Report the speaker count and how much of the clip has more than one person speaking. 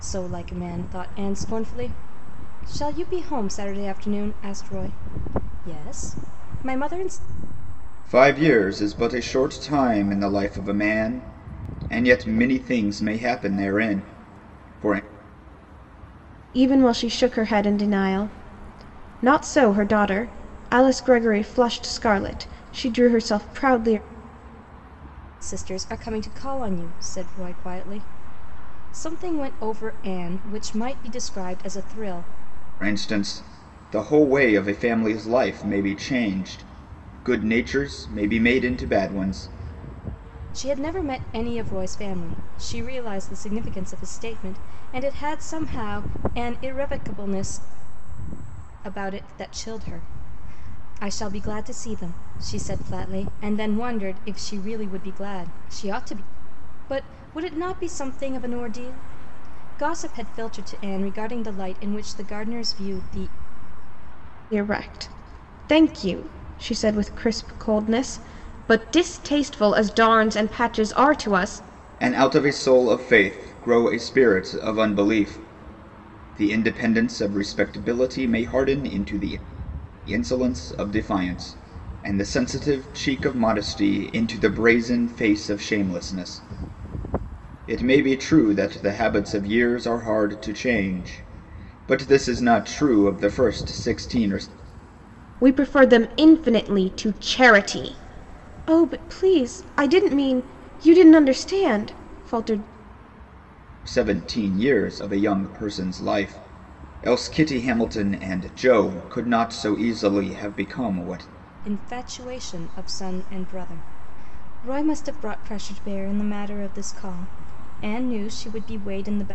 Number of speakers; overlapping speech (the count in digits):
3, no overlap